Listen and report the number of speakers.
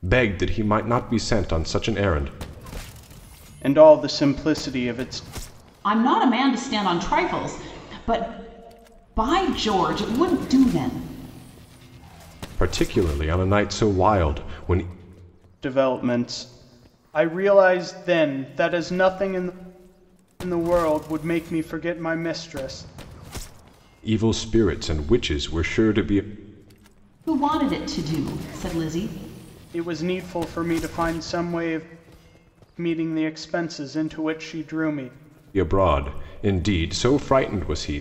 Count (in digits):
3